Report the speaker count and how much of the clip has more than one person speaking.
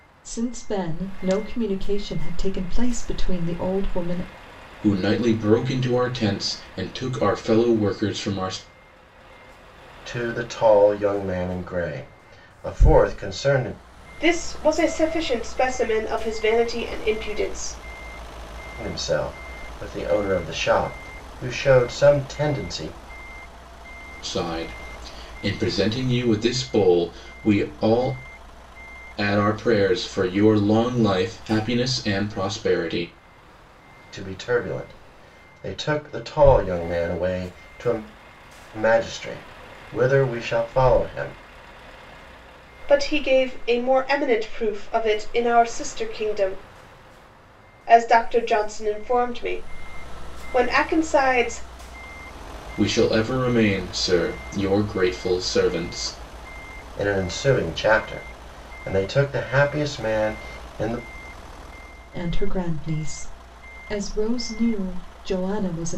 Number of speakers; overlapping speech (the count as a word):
four, no overlap